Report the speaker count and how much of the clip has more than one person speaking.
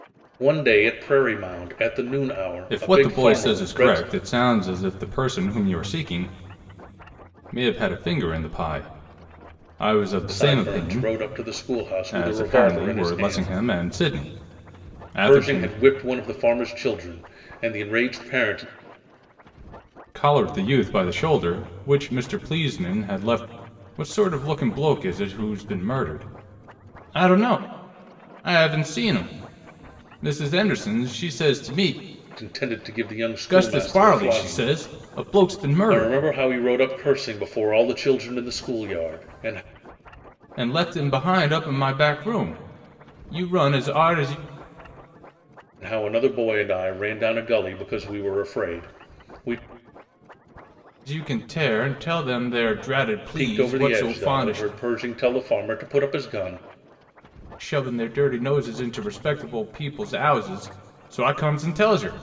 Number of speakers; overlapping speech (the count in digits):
2, about 12%